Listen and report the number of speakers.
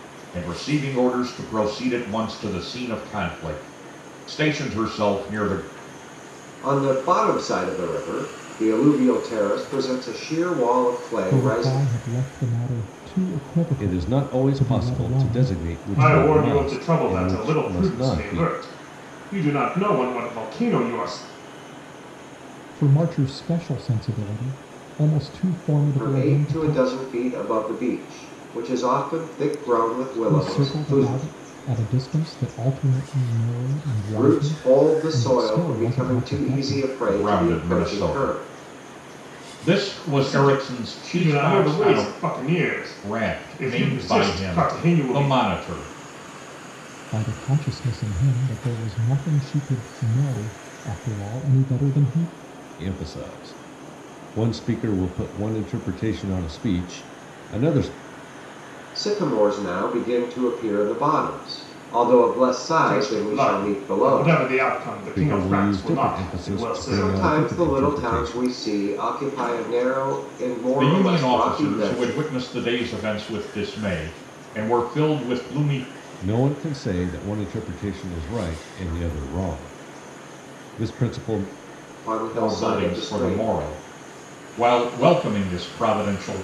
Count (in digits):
5